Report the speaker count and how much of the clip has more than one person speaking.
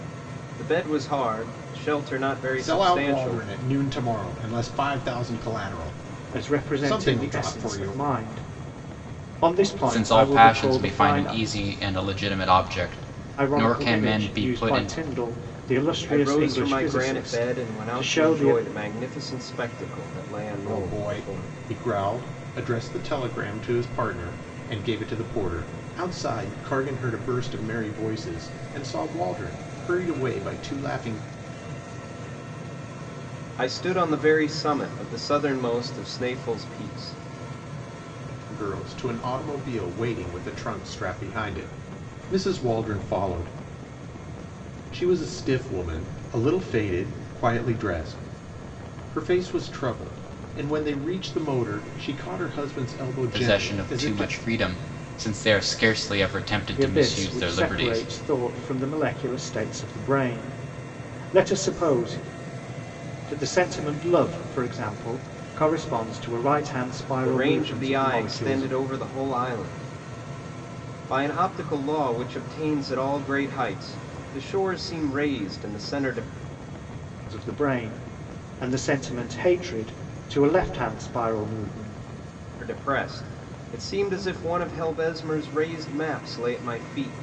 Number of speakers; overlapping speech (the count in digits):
4, about 15%